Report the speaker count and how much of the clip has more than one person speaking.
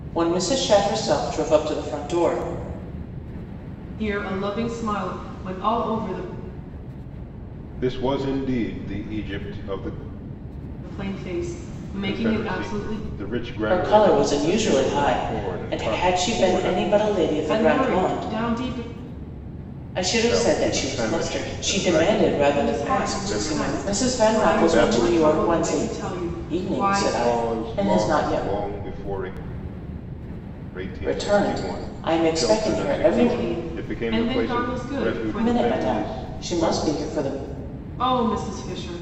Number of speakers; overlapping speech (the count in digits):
3, about 48%